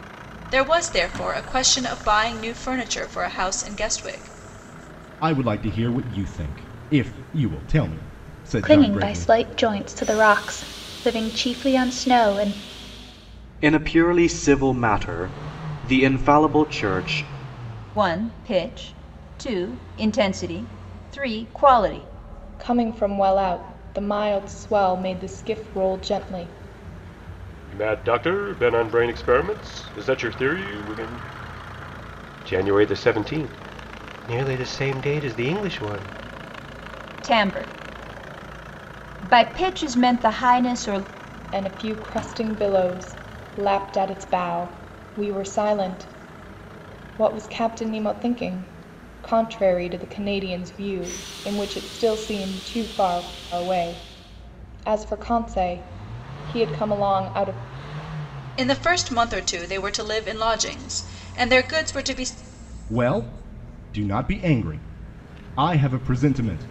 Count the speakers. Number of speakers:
seven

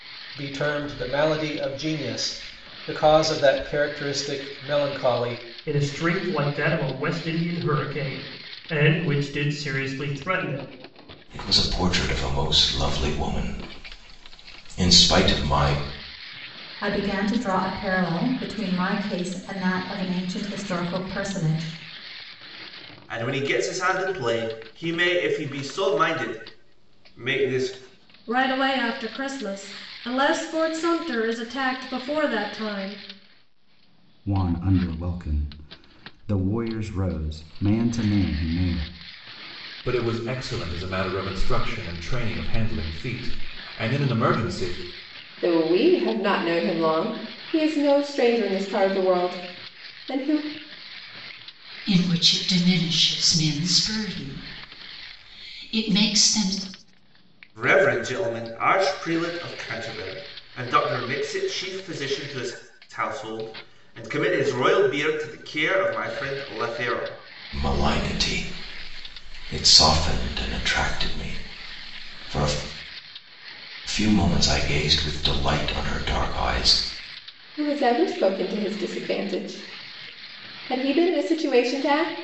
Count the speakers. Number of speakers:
ten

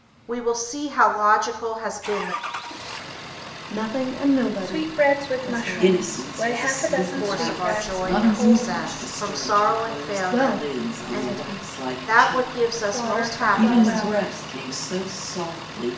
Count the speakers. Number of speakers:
four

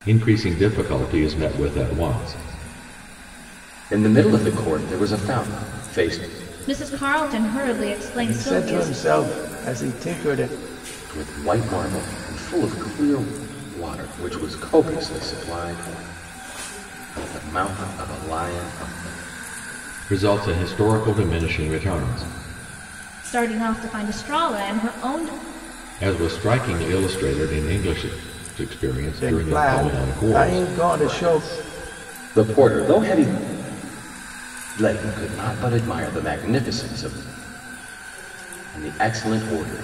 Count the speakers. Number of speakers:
four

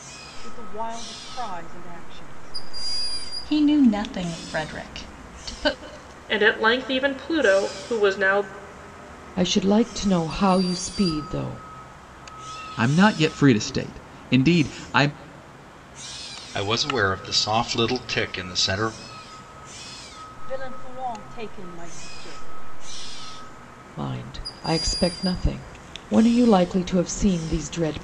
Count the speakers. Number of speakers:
six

